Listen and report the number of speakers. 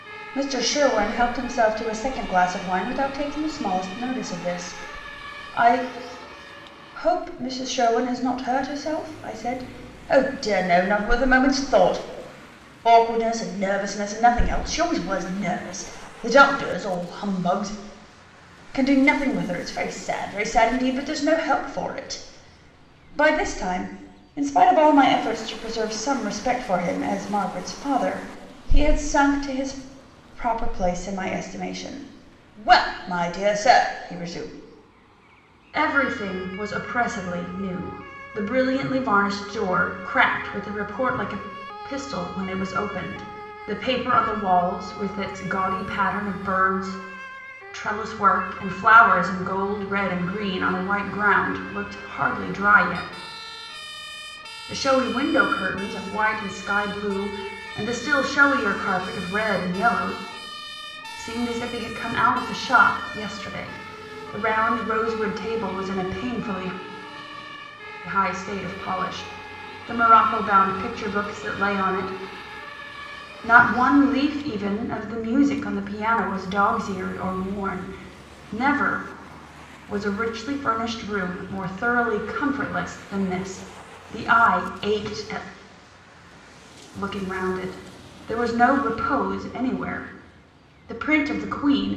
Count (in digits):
1